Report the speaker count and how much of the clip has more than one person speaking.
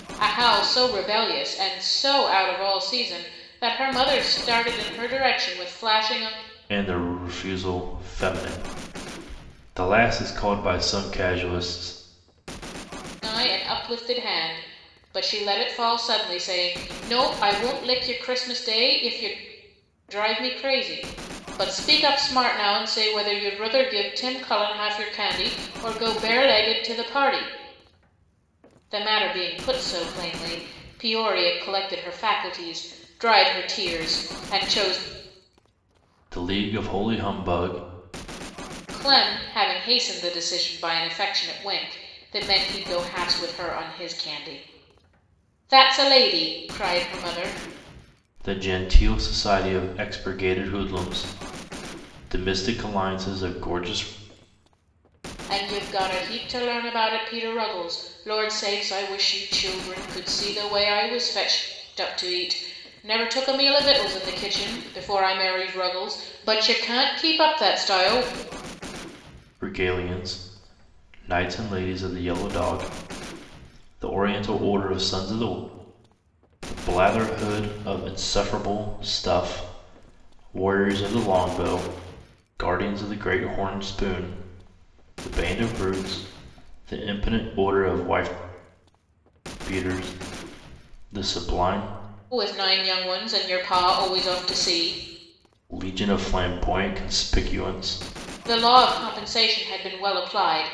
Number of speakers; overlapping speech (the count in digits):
2, no overlap